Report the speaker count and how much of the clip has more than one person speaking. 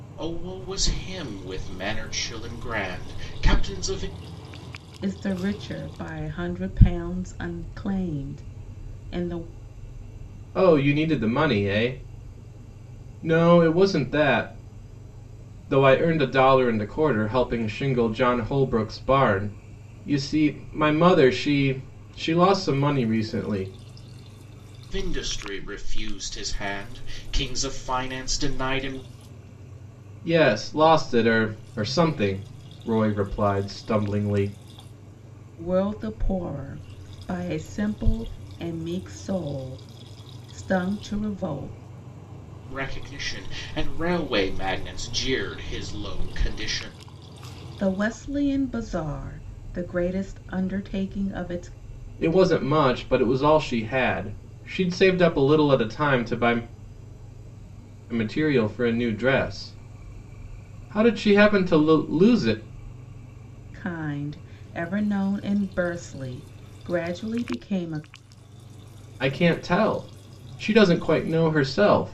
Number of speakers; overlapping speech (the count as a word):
three, no overlap